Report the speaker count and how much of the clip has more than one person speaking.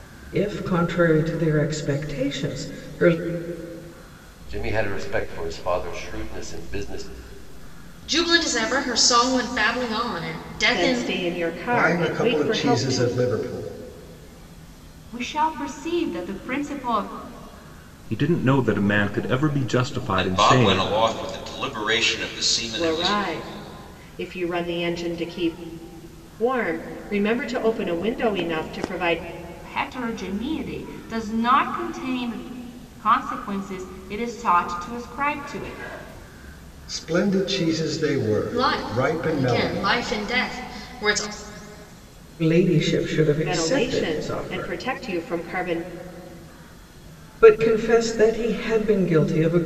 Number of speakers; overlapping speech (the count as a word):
eight, about 12%